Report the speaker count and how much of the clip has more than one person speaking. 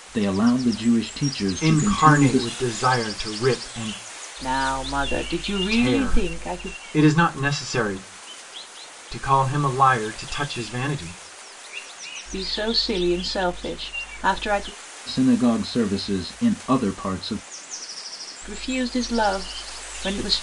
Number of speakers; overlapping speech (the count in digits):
3, about 10%